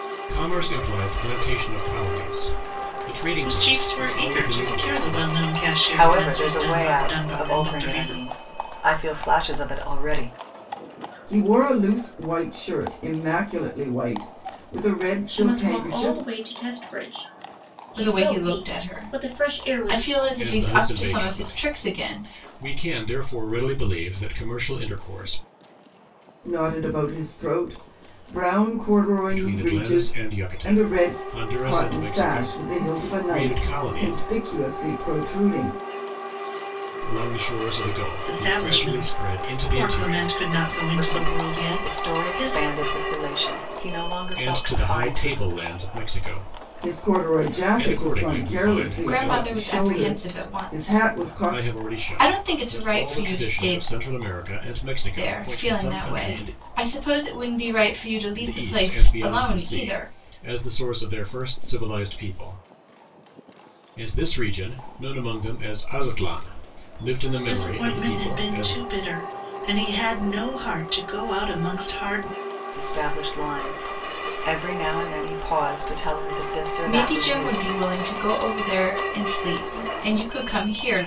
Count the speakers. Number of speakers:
six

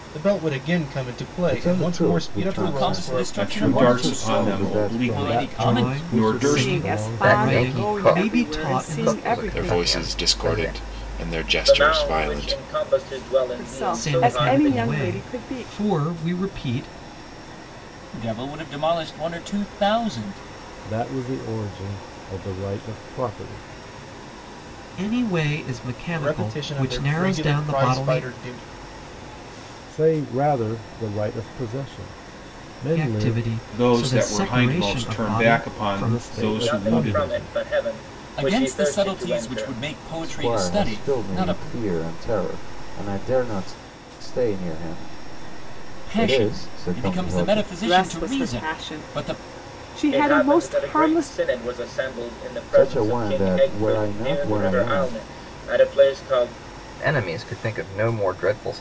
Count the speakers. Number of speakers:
ten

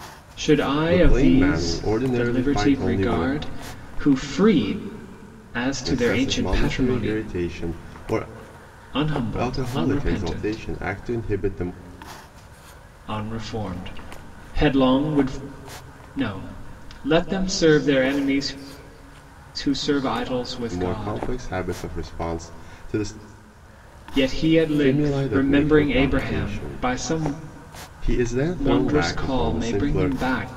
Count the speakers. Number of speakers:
two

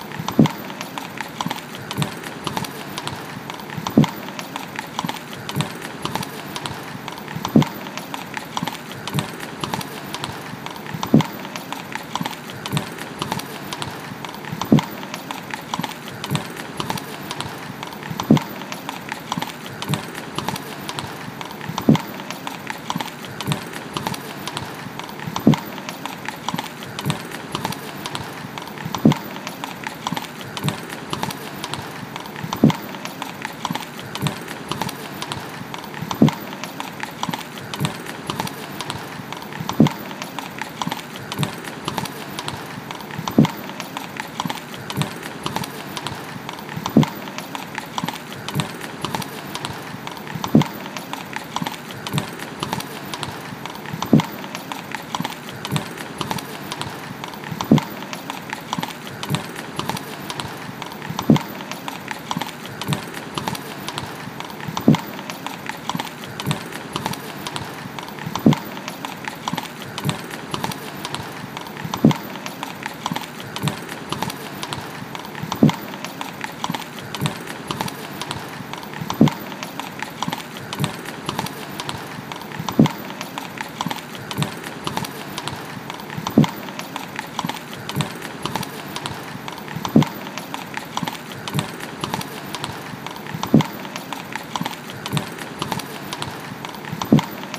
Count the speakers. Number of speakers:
zero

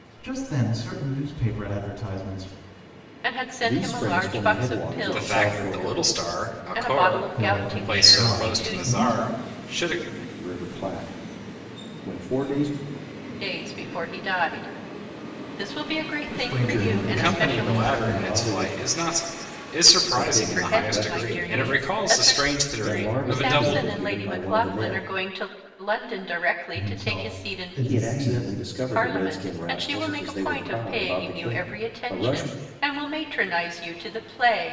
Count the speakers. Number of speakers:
four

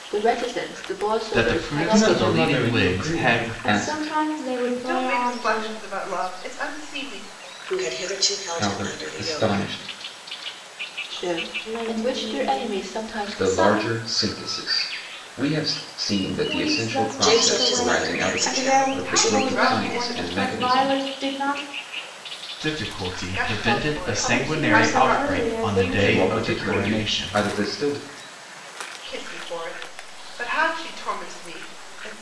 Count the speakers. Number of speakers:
six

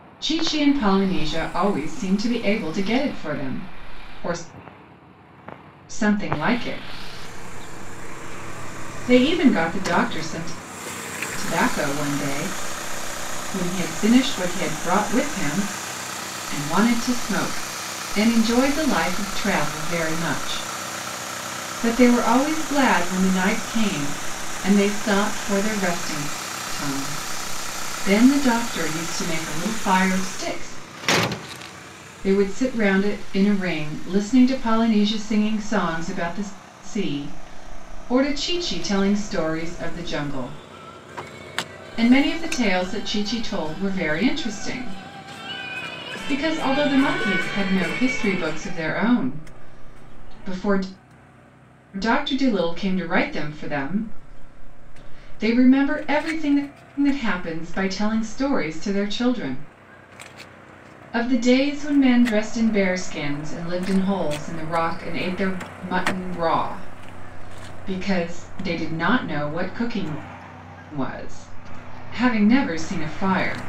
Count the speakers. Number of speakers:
one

